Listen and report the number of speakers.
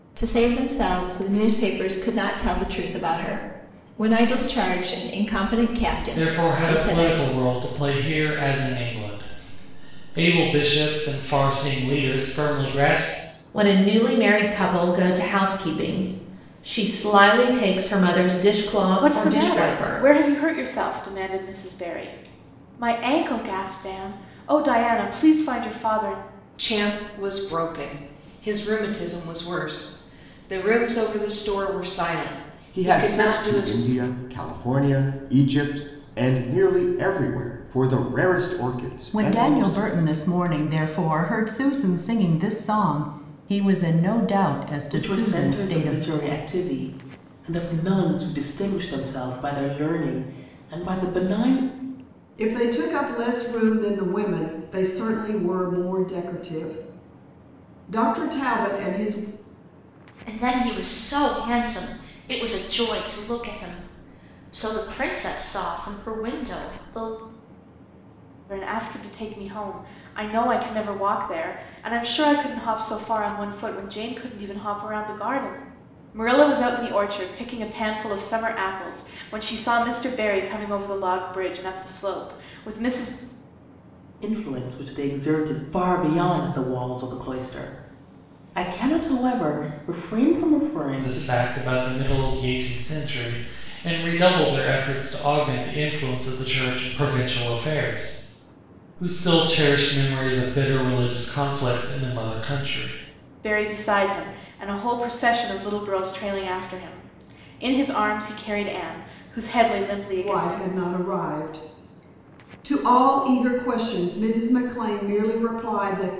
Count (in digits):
10